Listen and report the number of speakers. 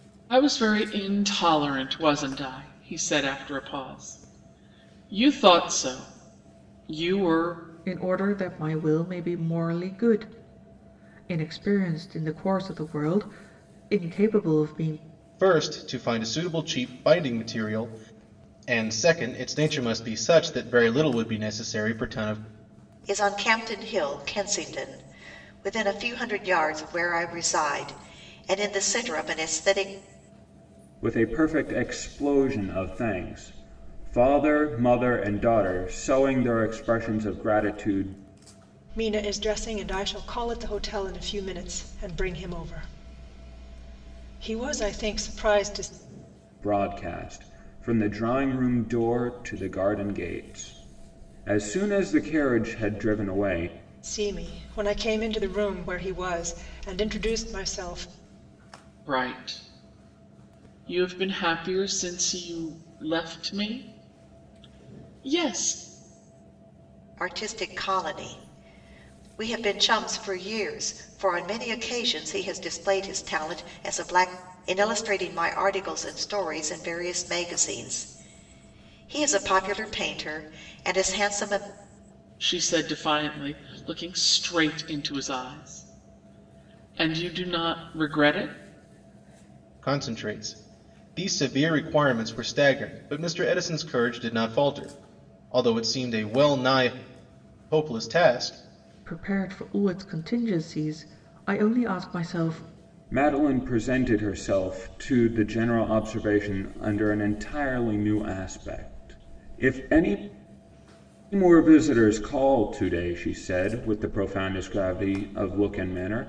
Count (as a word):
six